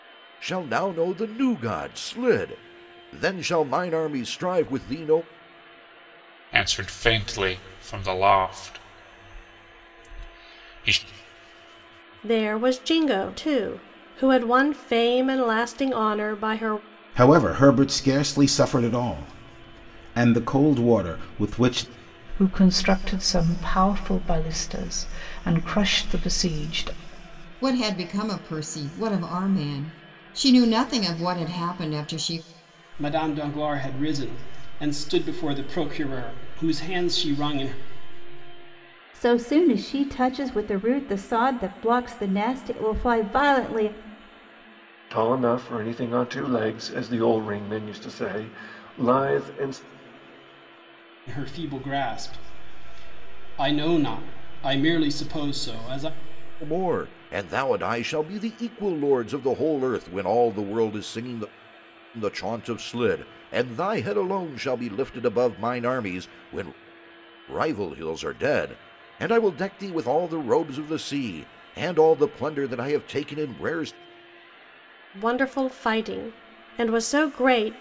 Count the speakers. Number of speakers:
9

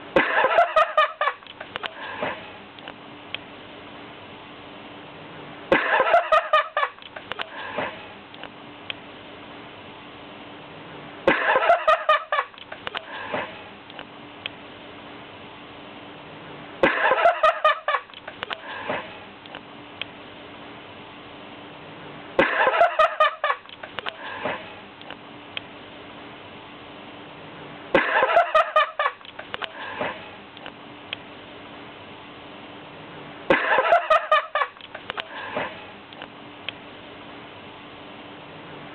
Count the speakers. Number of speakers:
0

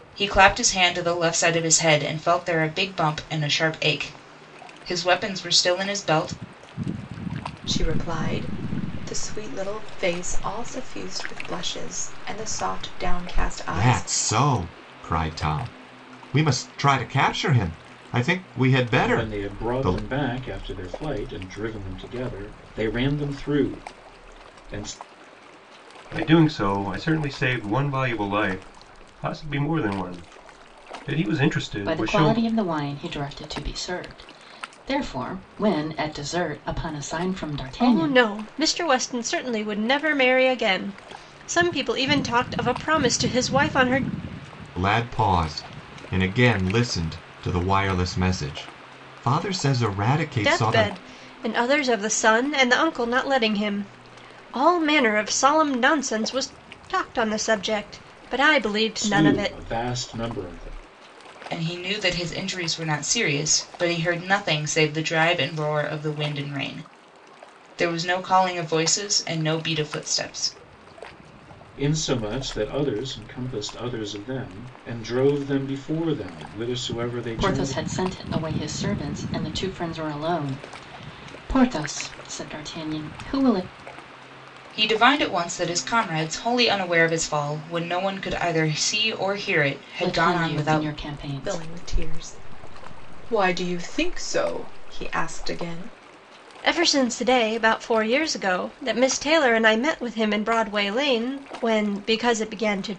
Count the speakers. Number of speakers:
7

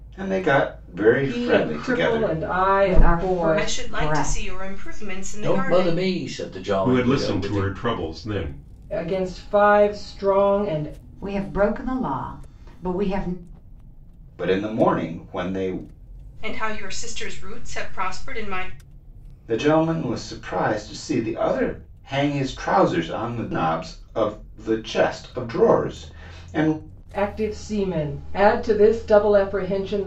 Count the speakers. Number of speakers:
6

